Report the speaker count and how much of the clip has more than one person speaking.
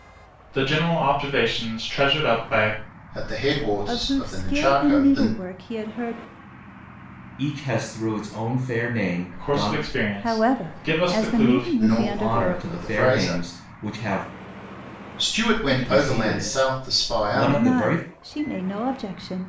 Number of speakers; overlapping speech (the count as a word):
four, about 38%